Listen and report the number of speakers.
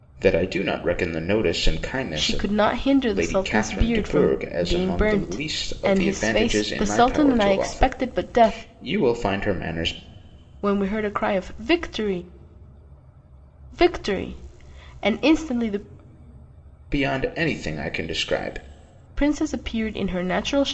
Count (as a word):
two